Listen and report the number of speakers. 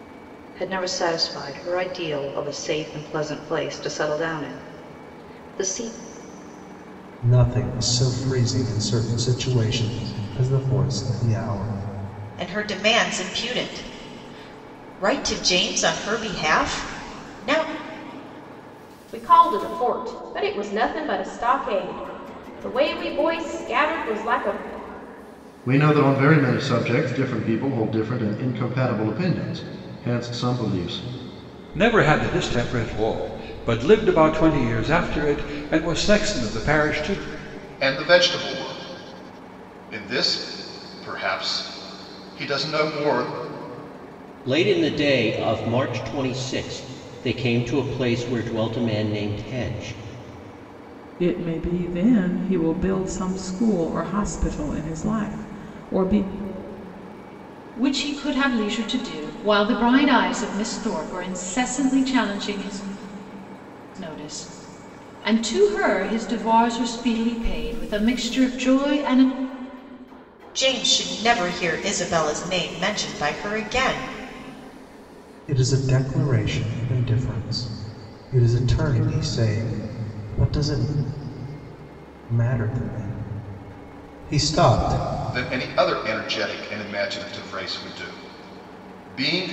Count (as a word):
ten